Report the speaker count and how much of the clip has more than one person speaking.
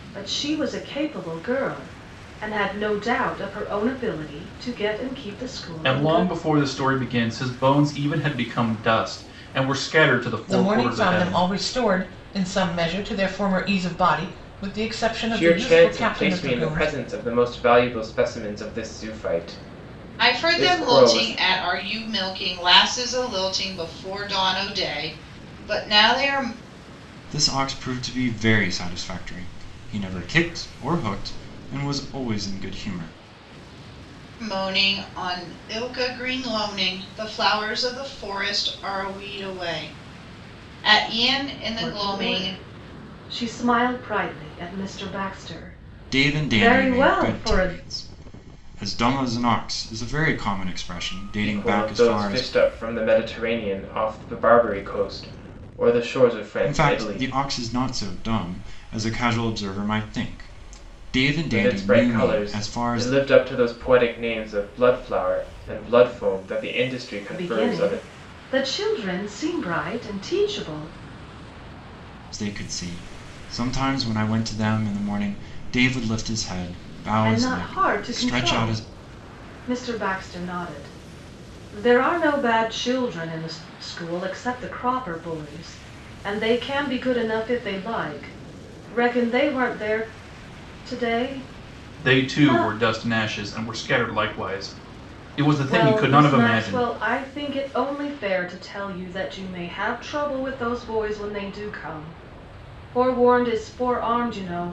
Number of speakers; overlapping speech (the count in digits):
6, about 14%